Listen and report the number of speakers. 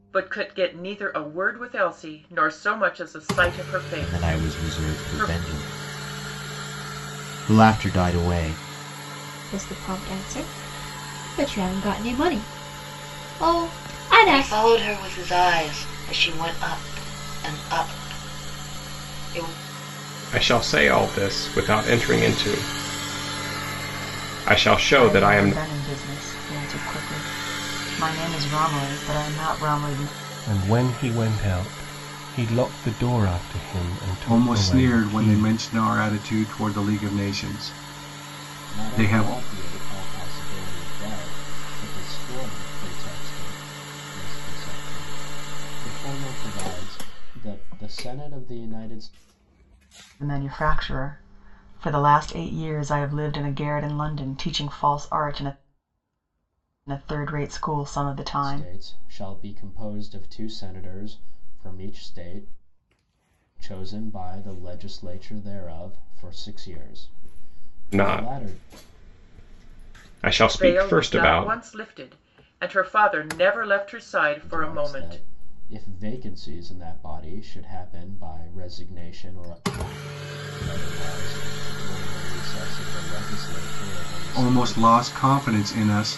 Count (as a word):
nine